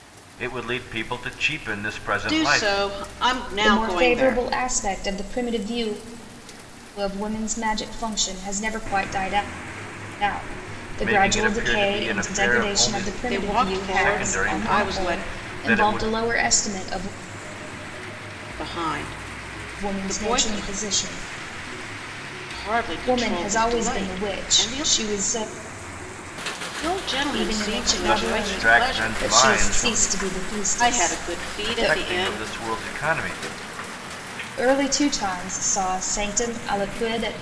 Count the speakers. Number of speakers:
three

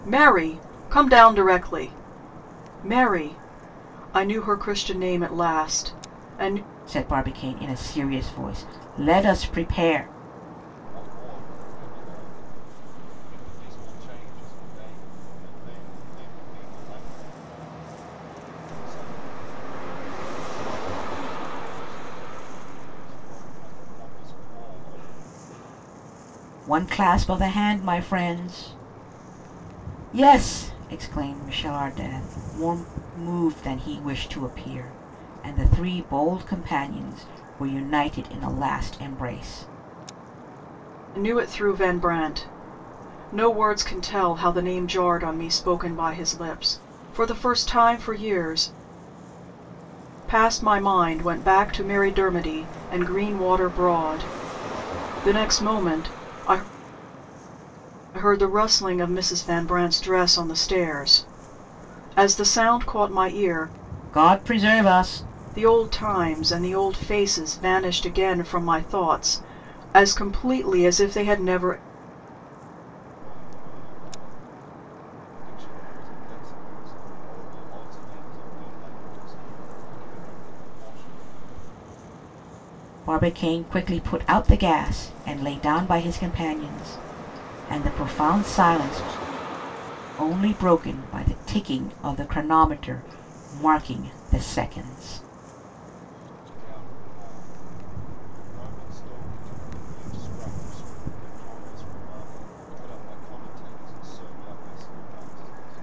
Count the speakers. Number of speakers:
three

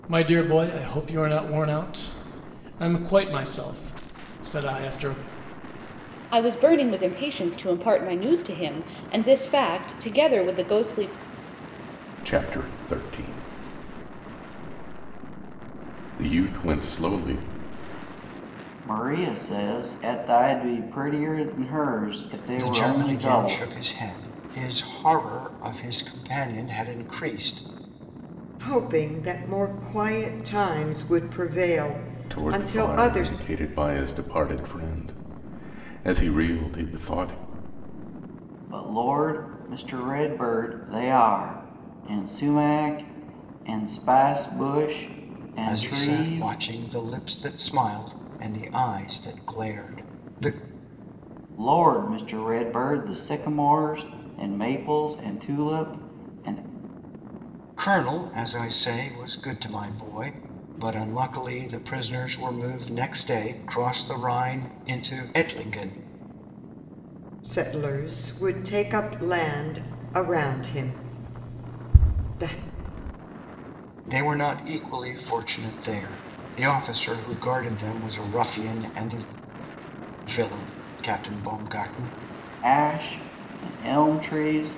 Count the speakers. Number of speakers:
six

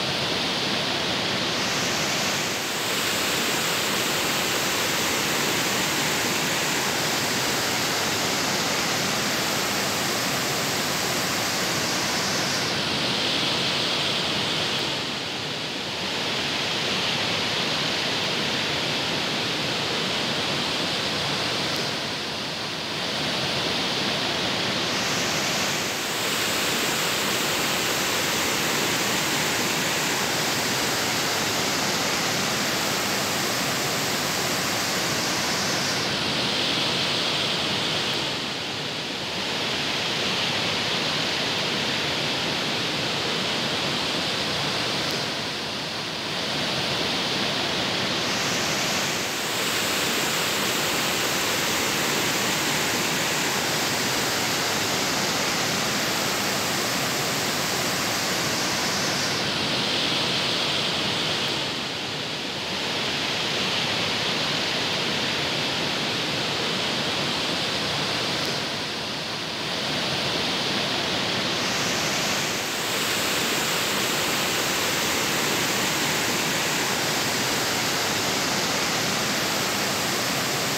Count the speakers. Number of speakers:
zero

